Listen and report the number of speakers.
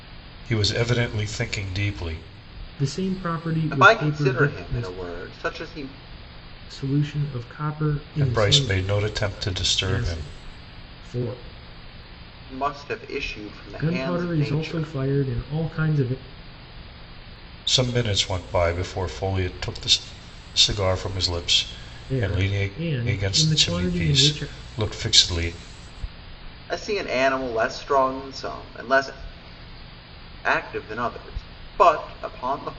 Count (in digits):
3